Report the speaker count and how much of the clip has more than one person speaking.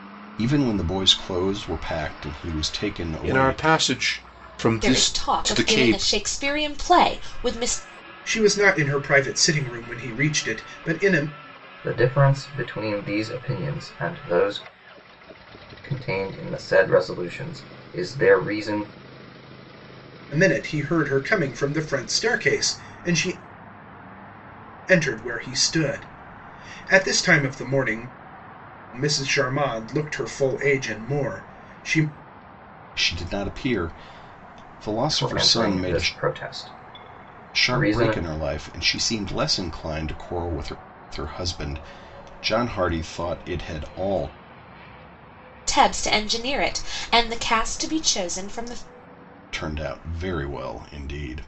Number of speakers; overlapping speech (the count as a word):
five, about 7%